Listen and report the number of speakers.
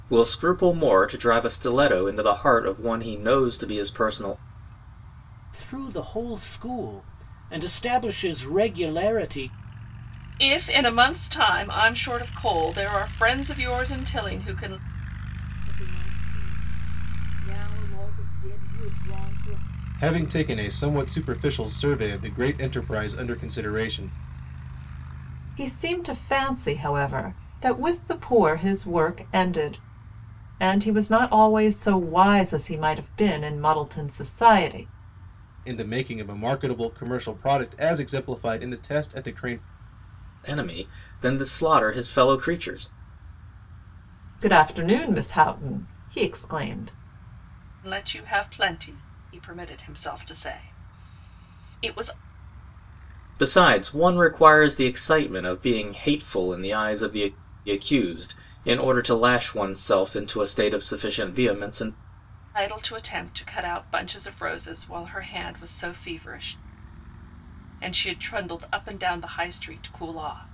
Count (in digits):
6